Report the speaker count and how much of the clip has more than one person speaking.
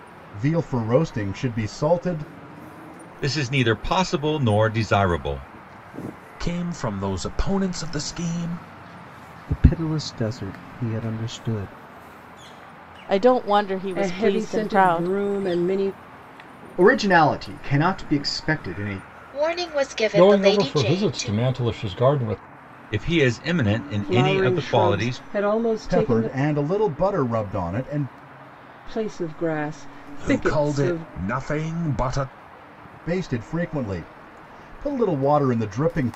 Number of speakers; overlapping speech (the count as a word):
nine, about 15%